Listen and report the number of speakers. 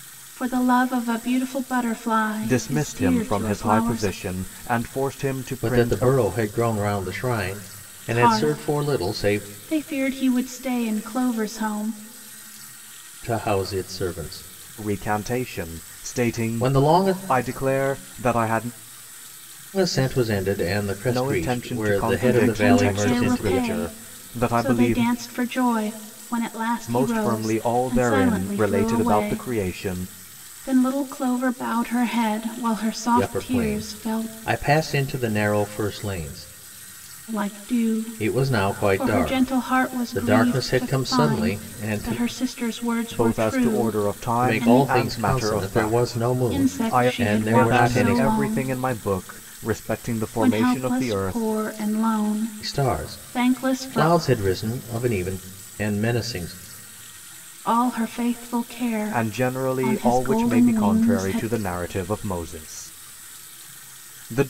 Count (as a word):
three